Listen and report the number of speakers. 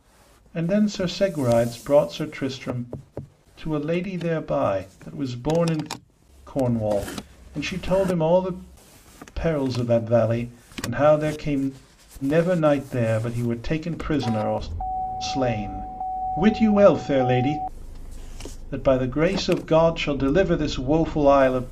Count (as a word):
one